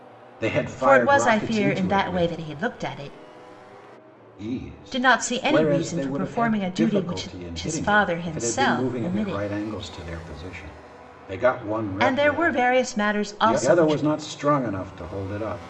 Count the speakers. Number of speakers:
2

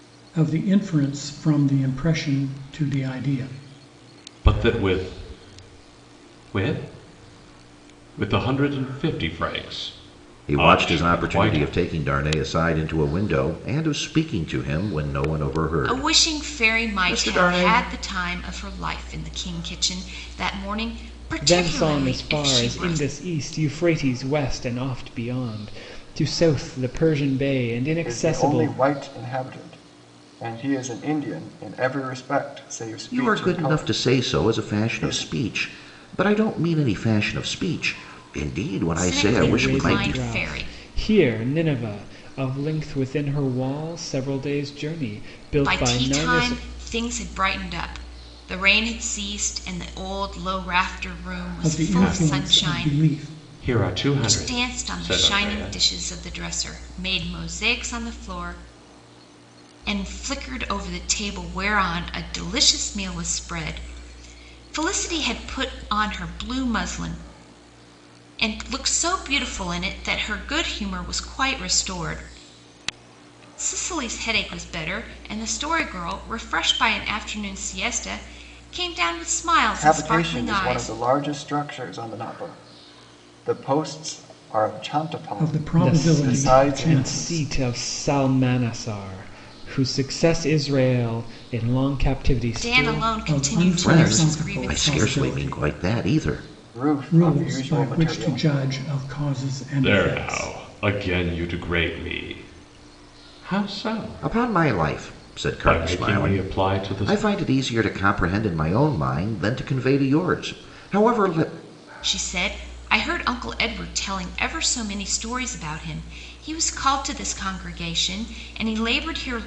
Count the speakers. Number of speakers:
6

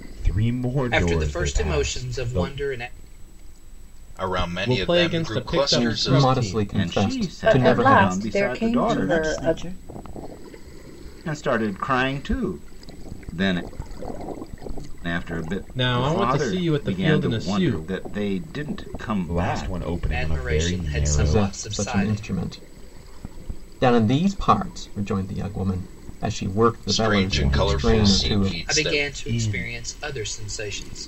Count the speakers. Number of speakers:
8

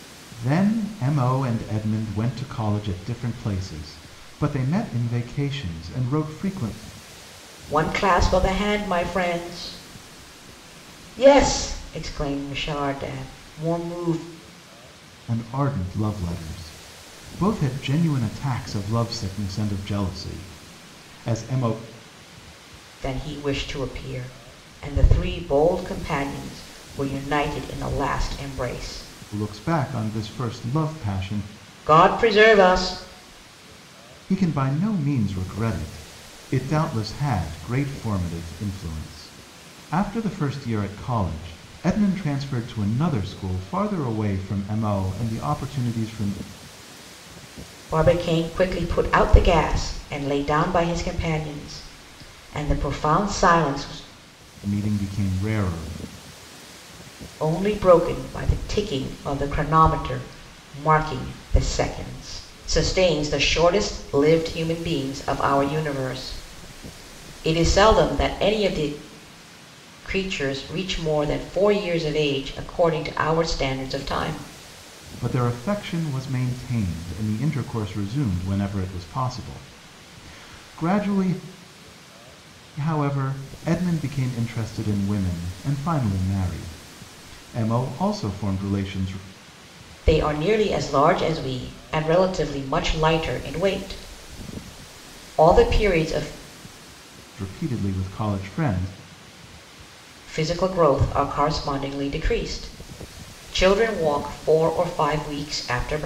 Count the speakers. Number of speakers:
2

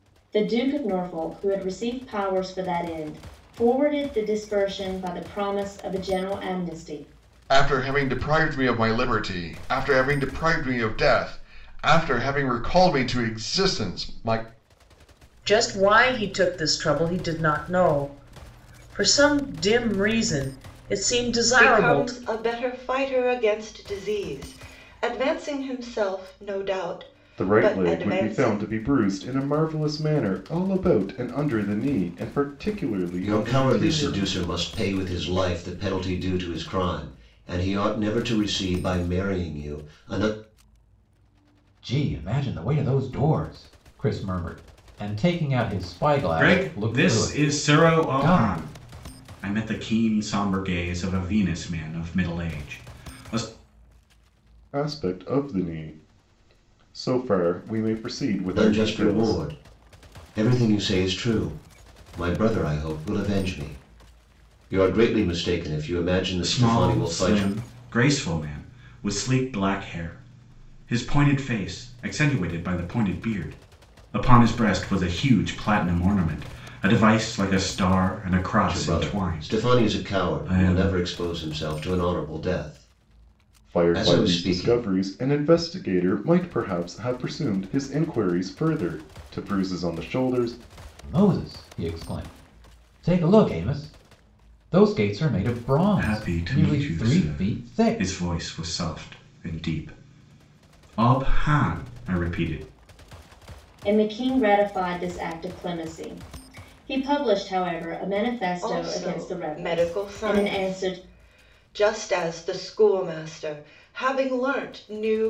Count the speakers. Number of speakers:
8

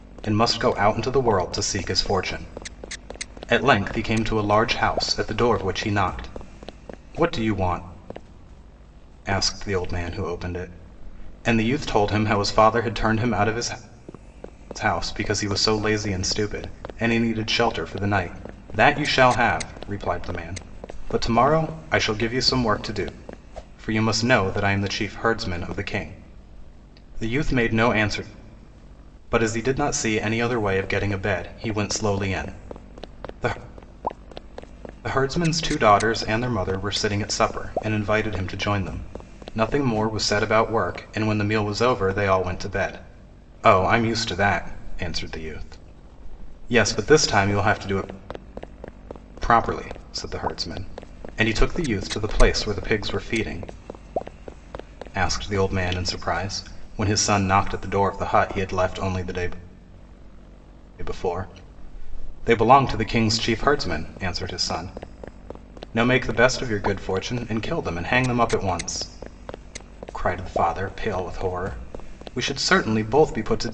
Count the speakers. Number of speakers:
1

